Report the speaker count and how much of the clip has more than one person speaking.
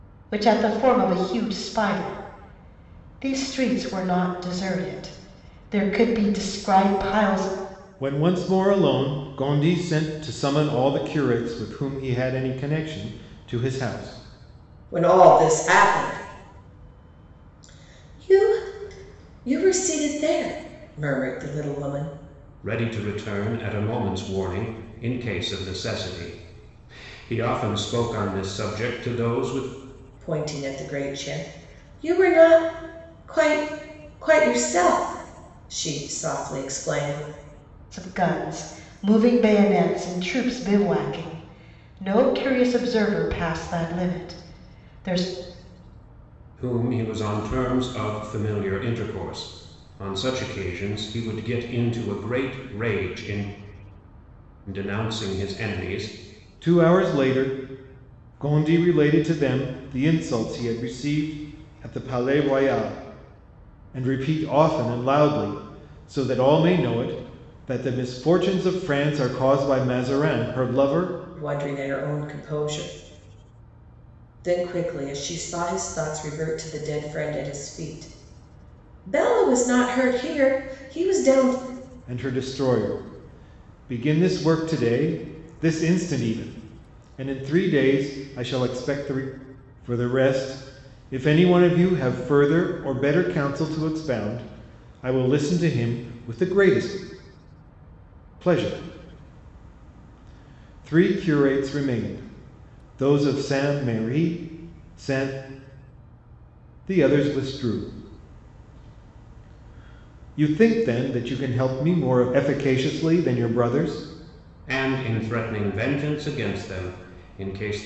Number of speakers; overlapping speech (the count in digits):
4, no overlap